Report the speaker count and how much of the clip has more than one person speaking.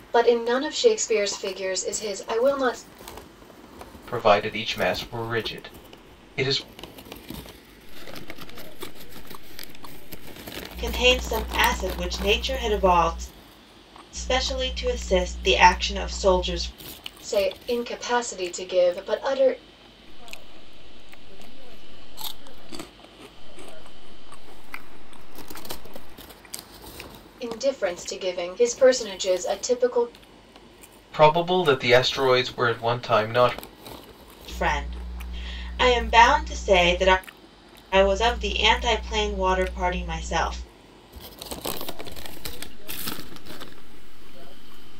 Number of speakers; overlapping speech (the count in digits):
4, no overlap